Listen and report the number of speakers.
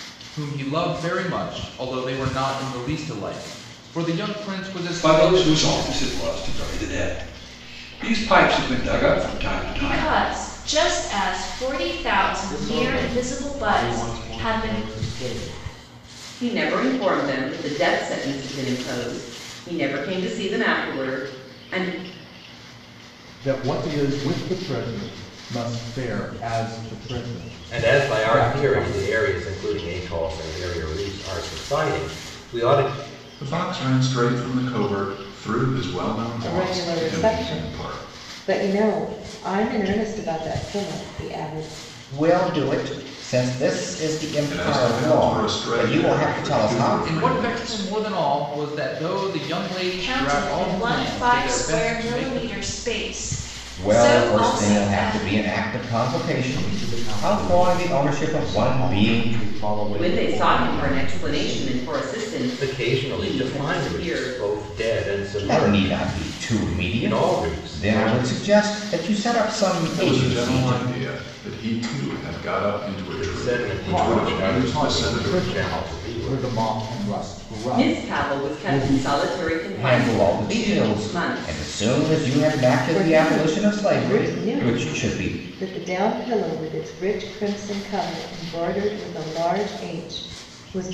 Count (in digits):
10